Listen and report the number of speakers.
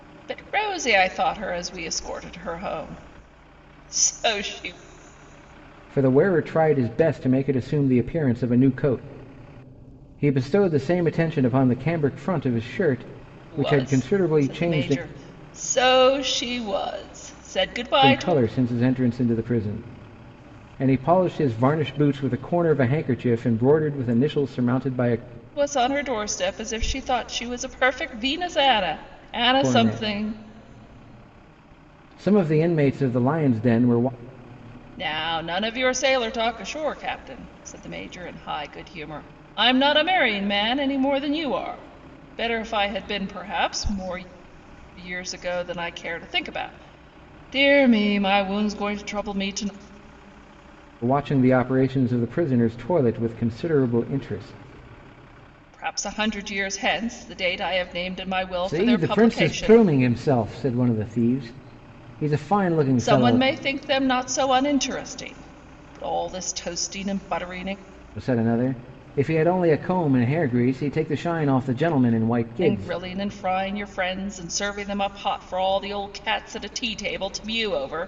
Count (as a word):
two